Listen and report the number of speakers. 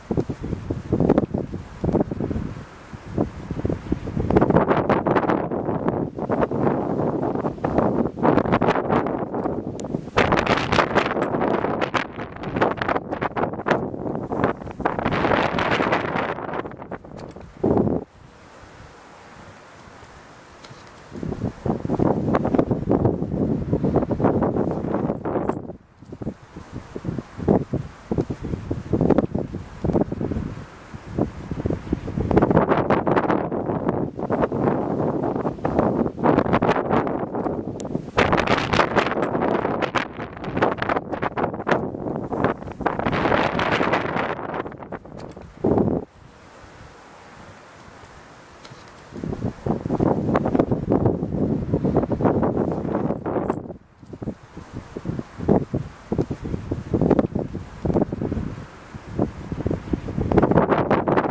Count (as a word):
zero